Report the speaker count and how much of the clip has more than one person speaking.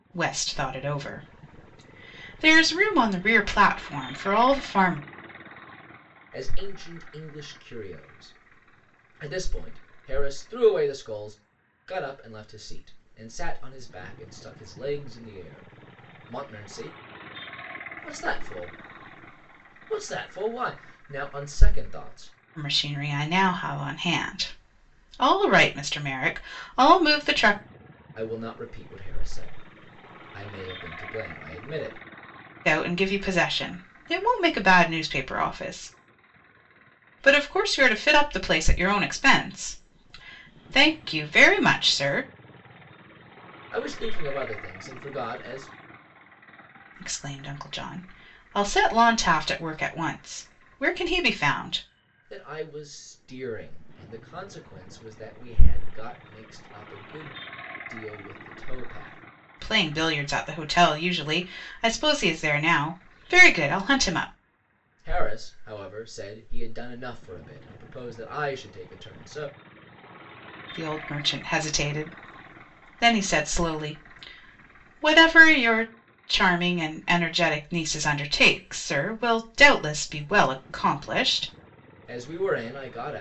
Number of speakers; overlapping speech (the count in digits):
2, no overlap